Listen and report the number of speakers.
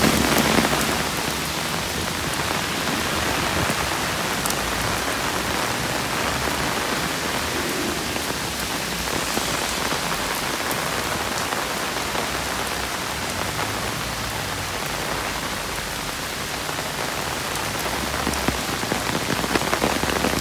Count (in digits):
0